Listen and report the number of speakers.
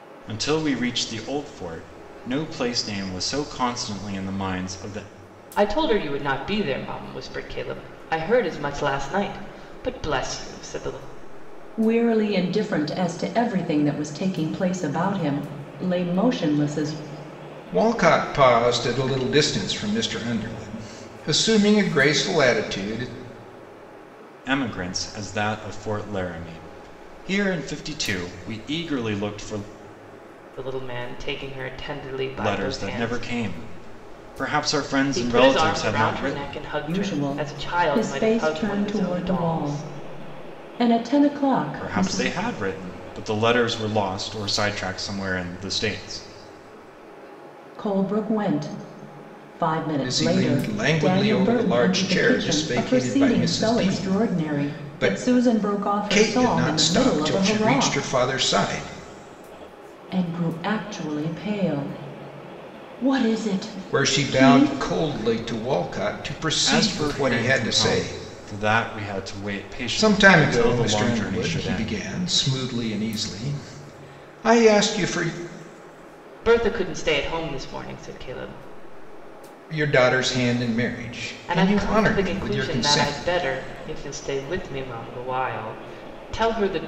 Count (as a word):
four